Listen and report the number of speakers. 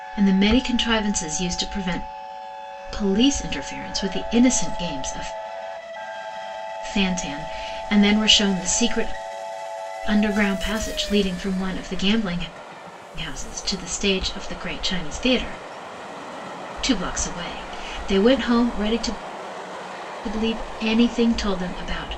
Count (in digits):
1